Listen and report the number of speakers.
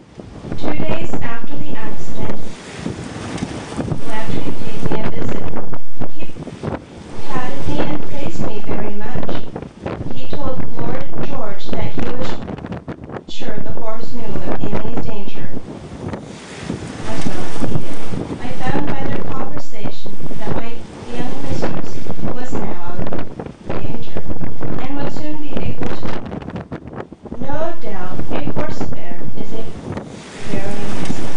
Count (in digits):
1